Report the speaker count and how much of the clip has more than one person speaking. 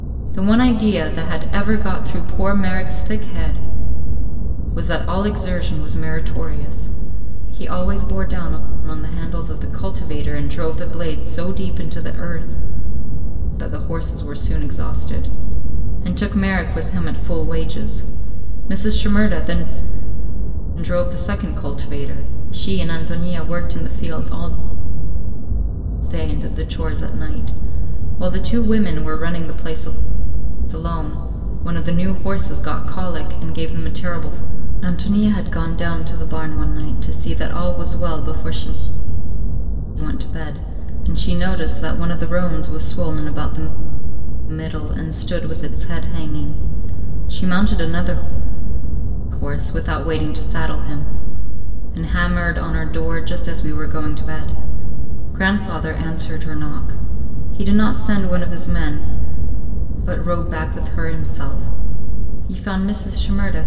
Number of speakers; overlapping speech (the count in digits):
1, no overlap